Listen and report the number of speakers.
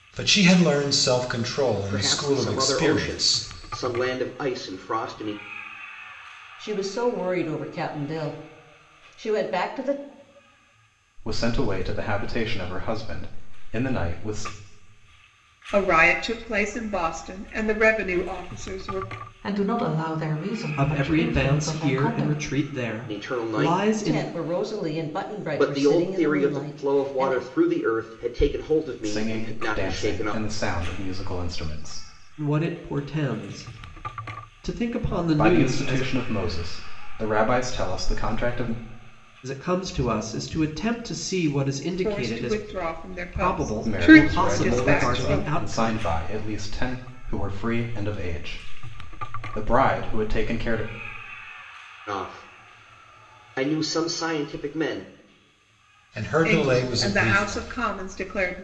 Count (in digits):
7